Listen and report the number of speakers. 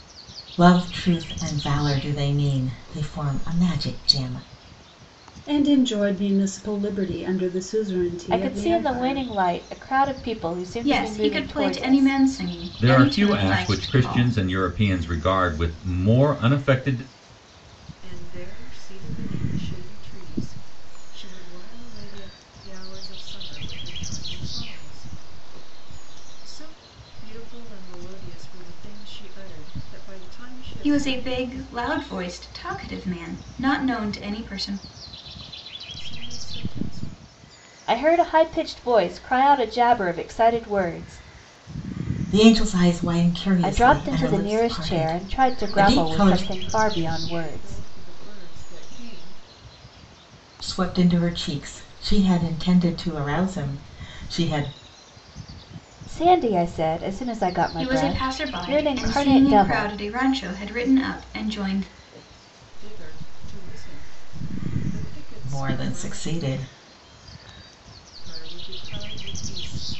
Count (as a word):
six